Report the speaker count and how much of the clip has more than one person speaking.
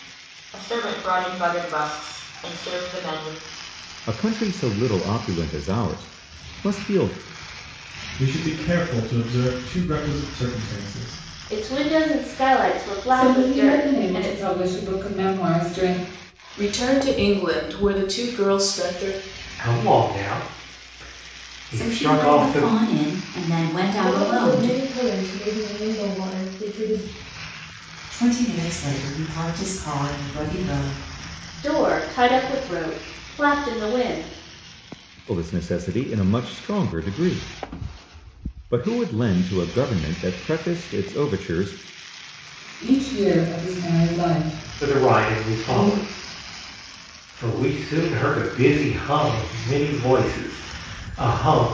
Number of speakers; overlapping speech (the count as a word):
ten, about 8%